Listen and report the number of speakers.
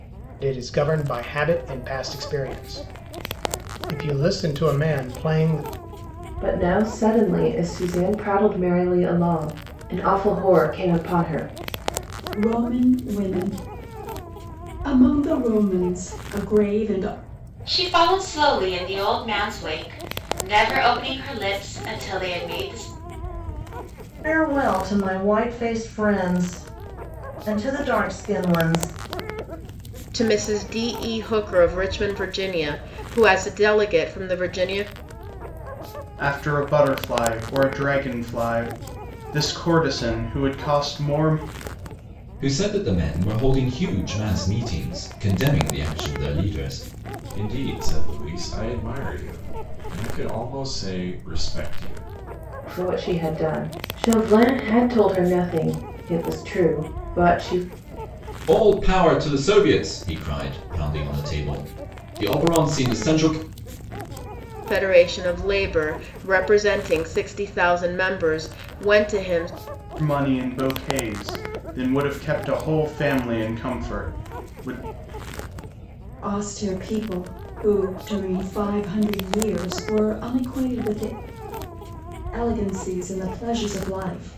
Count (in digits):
9